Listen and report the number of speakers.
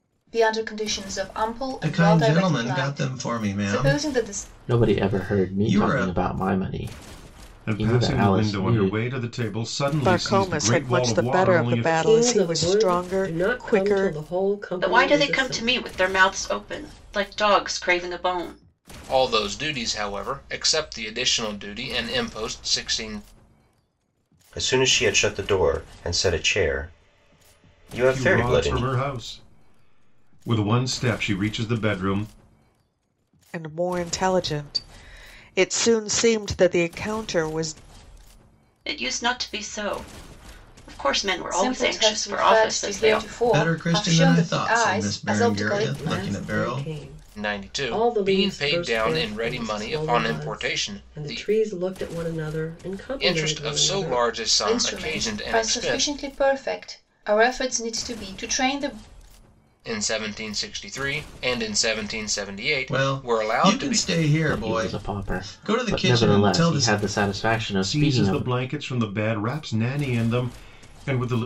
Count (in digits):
9